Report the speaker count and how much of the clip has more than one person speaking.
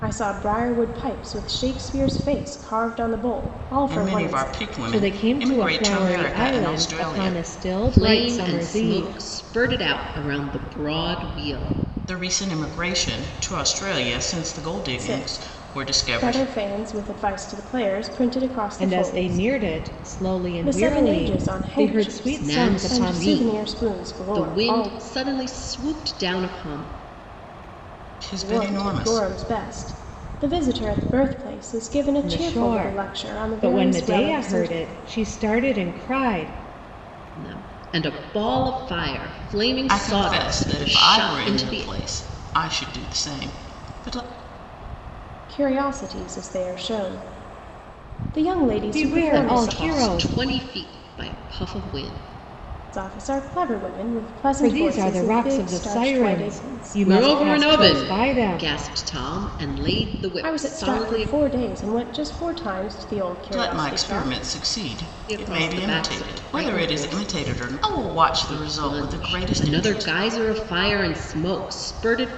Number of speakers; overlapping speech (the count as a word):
four, about 40%